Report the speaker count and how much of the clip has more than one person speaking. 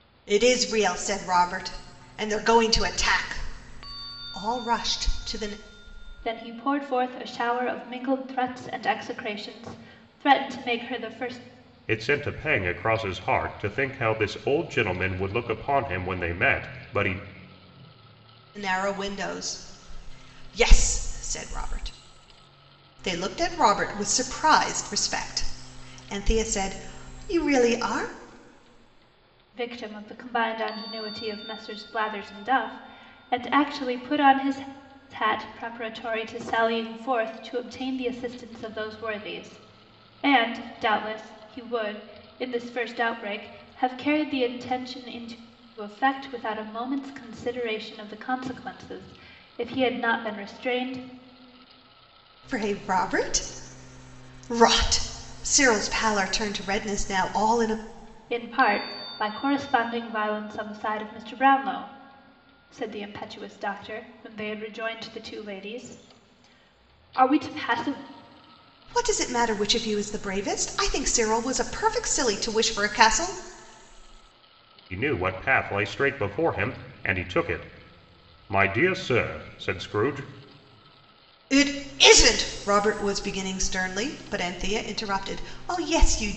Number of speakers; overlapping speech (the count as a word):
three, no overlap